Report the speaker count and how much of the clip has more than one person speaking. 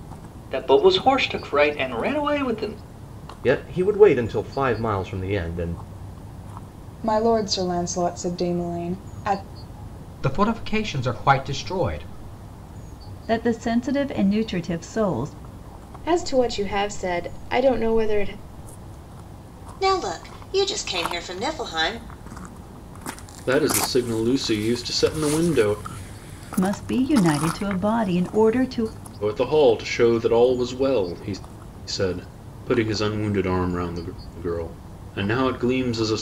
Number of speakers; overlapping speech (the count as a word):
eight, no overlap